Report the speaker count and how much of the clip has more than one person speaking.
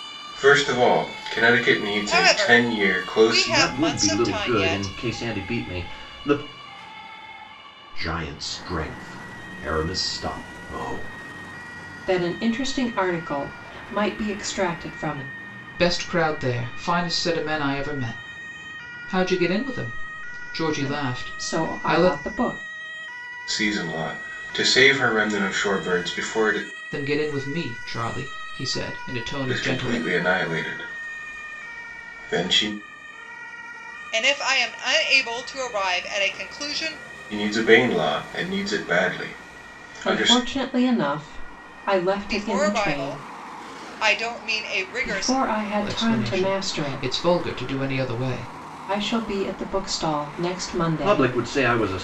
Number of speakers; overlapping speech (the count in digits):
6, about 16%